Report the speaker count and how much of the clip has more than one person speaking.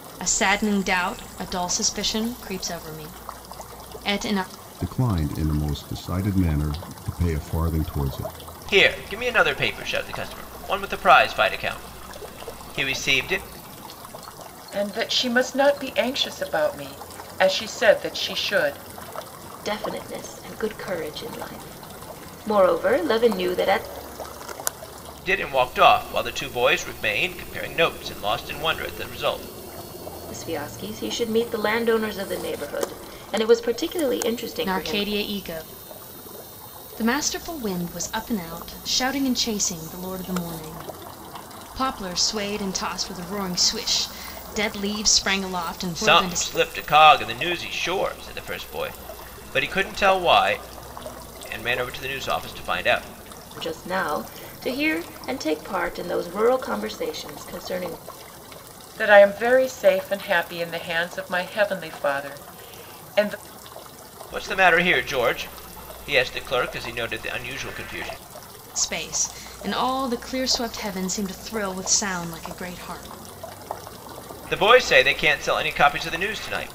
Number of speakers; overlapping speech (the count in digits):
5, about 1%